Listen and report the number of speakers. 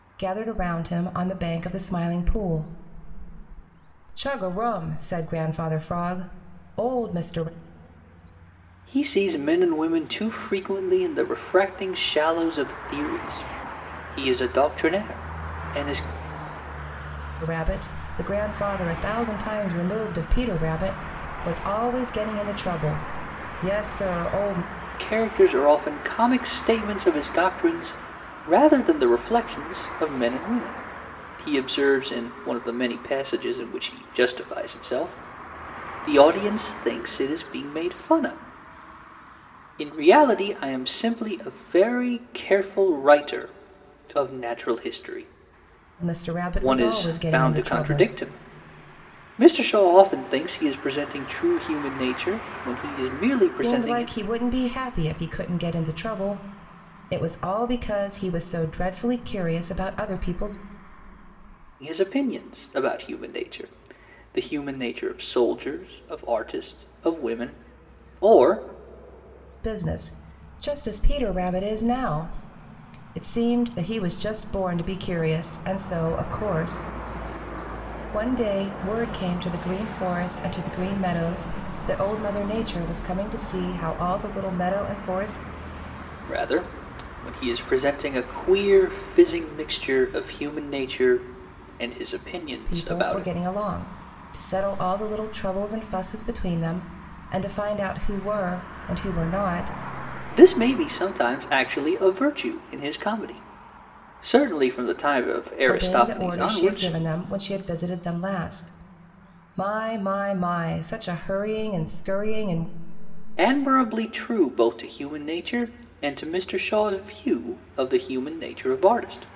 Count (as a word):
two